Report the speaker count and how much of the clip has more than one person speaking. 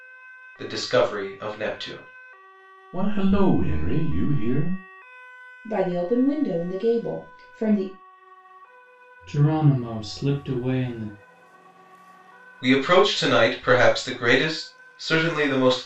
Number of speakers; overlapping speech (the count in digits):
4, no overlap